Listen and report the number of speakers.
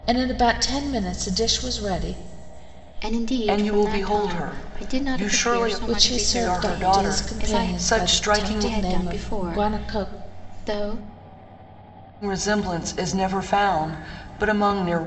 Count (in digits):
3